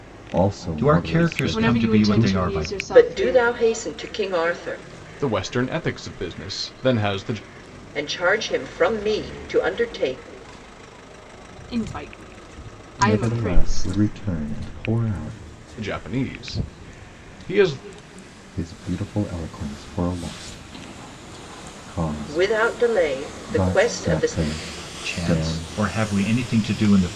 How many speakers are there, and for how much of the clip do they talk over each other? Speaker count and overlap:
5, about 23%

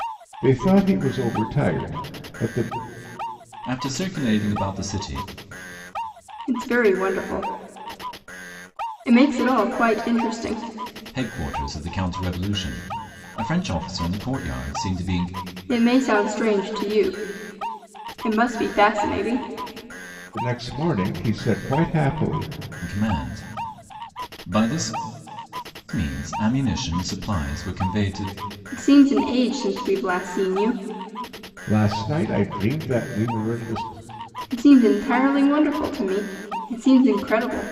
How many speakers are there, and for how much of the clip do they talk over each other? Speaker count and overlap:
3, no overlap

